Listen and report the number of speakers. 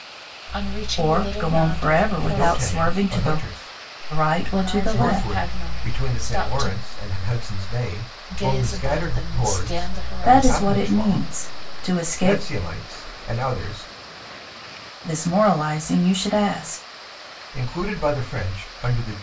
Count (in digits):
4